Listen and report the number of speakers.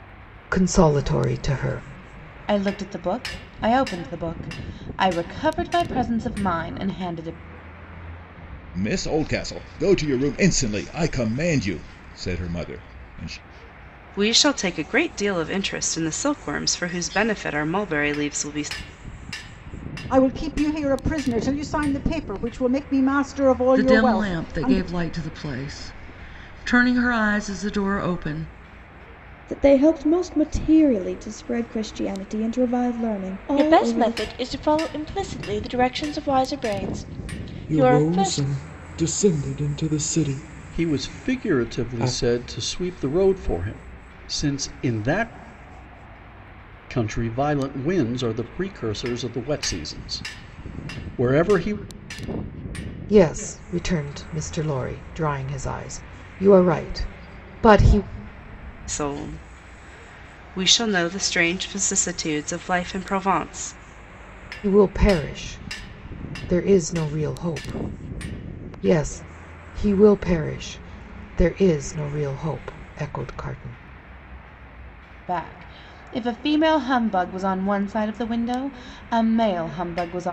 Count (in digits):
10